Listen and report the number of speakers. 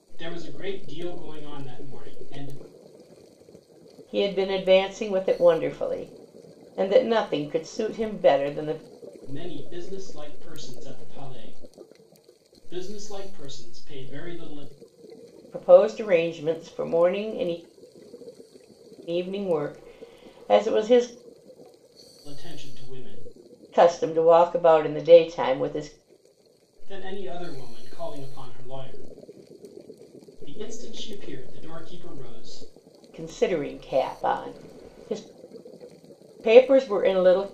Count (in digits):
2